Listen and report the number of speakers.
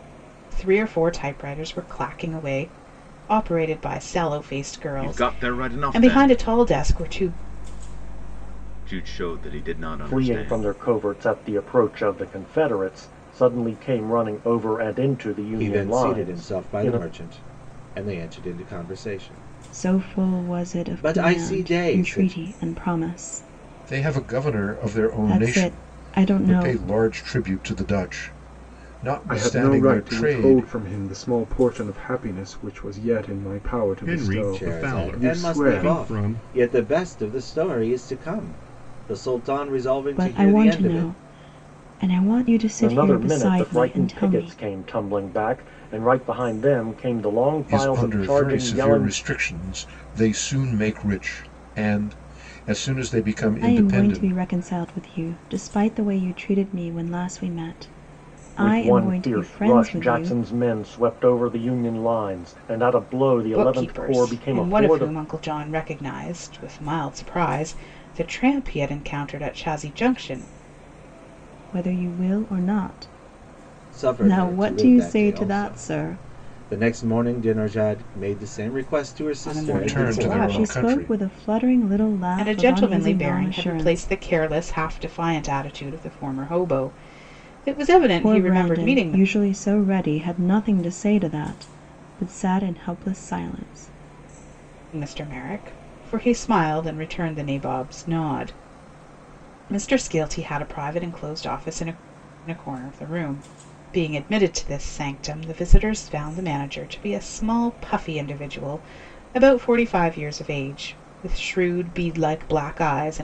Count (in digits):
8